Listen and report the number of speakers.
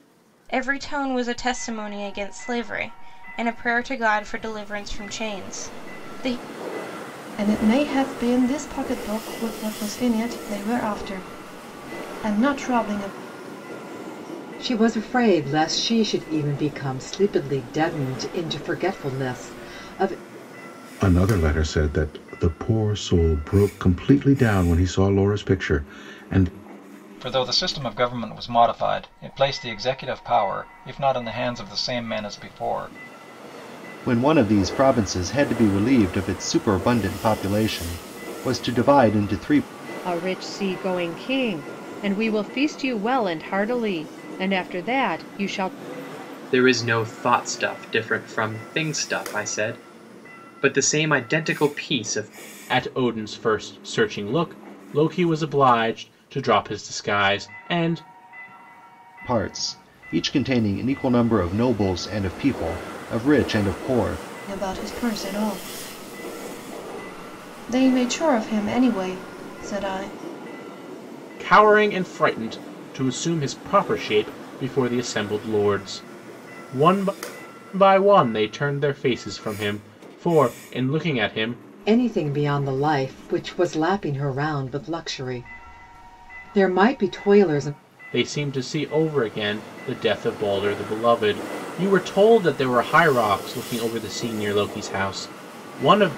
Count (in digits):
9